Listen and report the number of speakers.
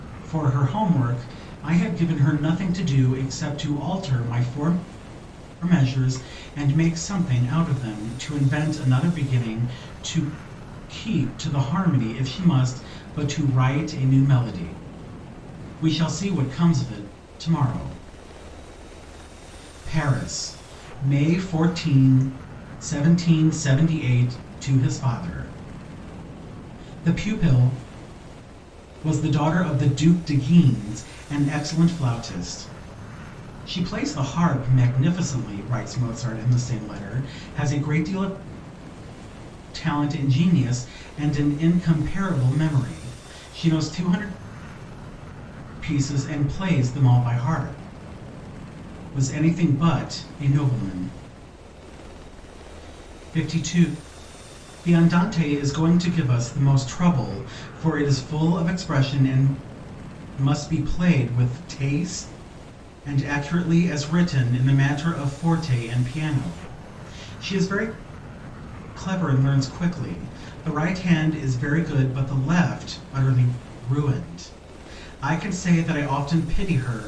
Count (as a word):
one